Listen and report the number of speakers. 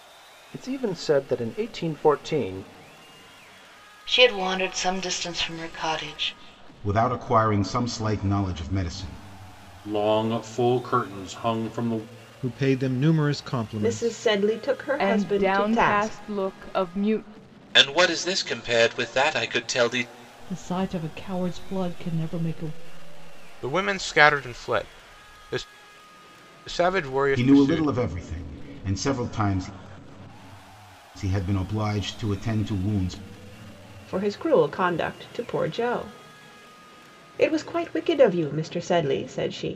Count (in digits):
10